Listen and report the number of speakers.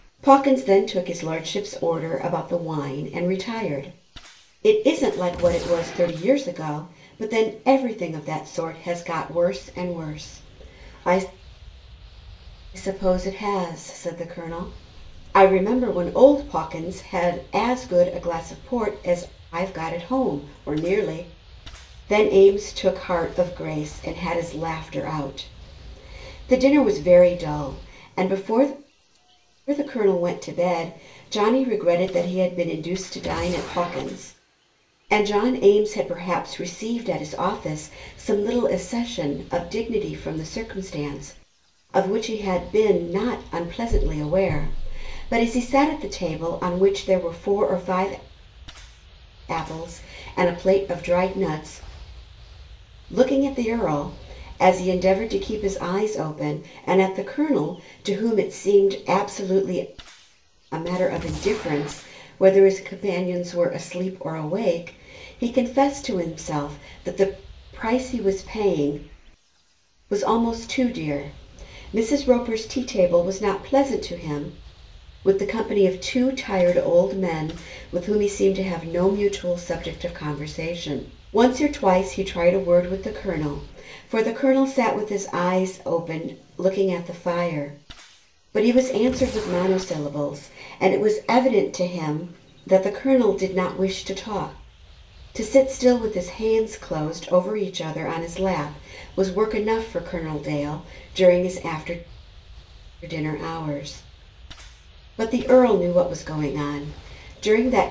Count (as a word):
one